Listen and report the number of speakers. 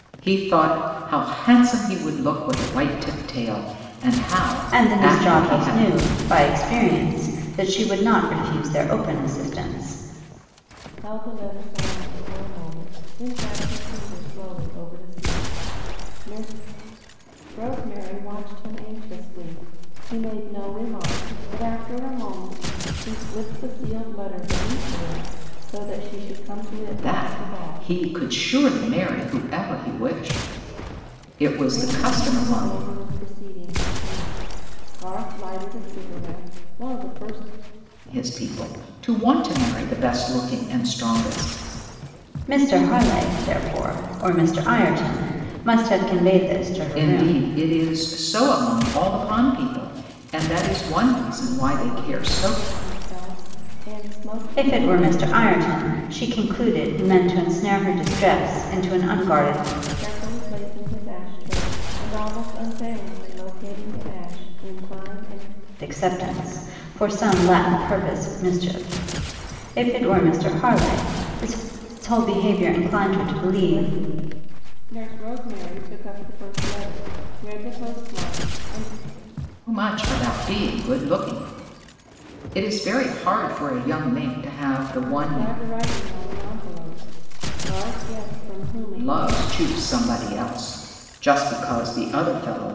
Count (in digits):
3